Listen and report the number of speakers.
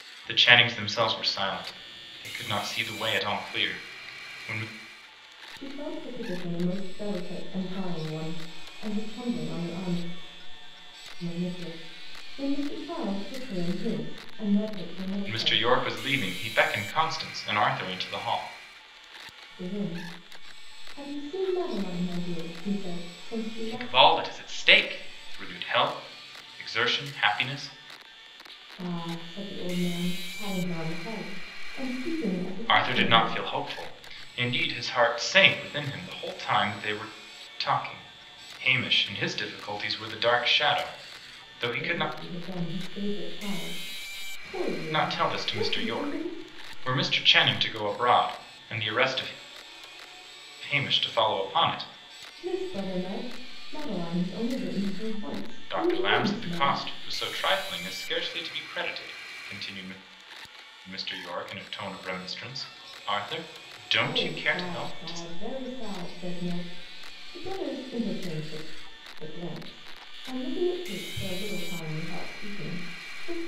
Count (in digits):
2